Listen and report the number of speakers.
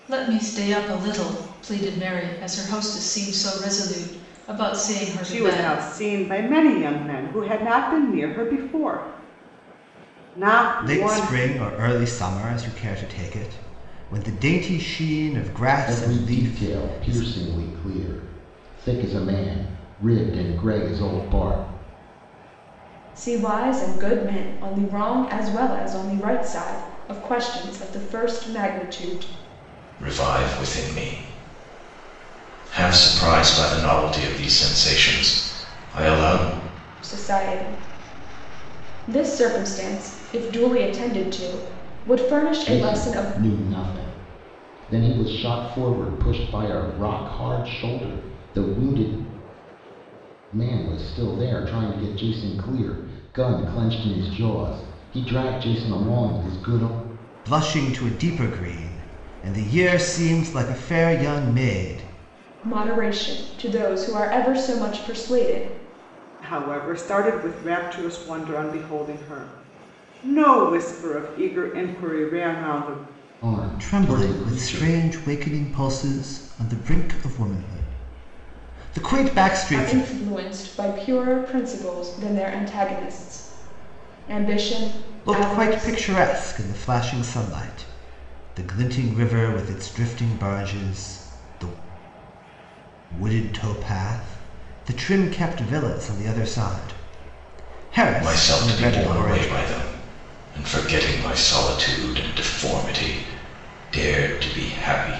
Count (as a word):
six